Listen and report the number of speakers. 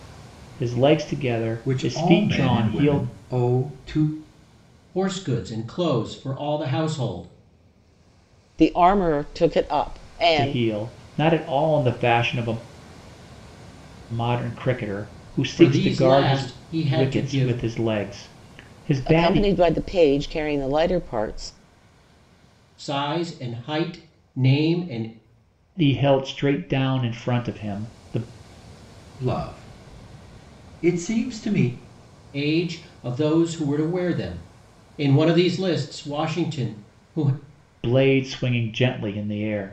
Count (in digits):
4